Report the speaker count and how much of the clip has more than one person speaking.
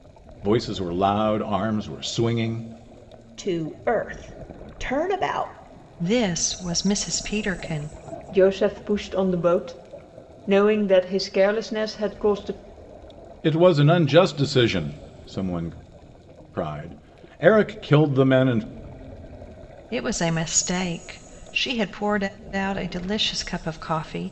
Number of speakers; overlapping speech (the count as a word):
four, no overlap